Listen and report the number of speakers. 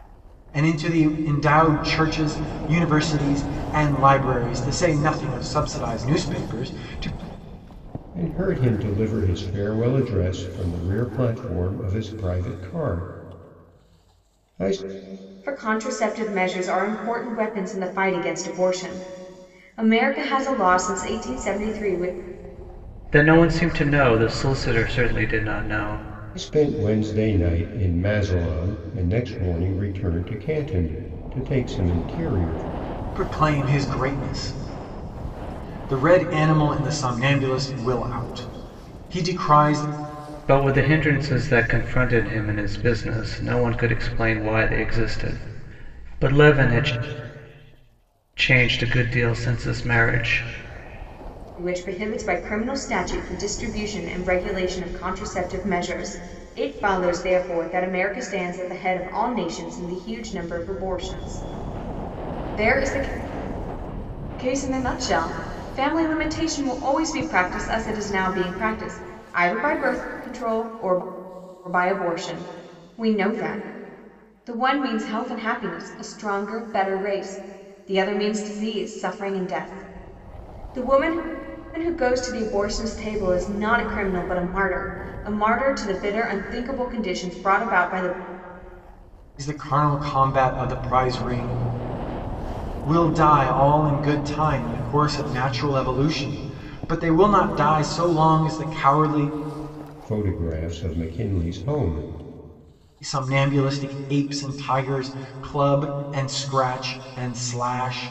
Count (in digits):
4